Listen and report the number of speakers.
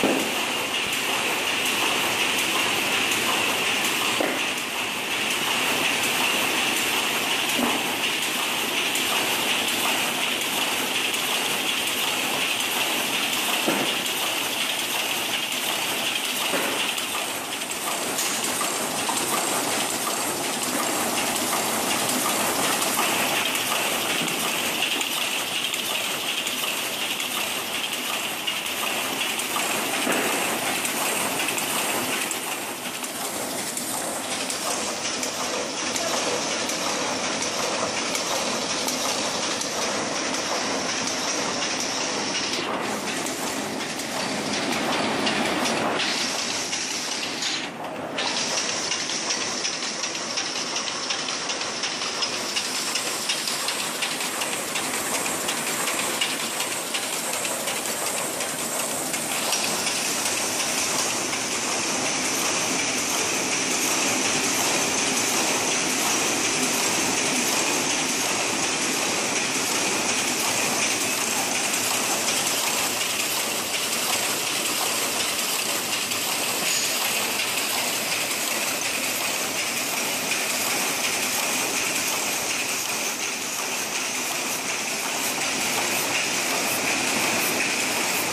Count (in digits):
0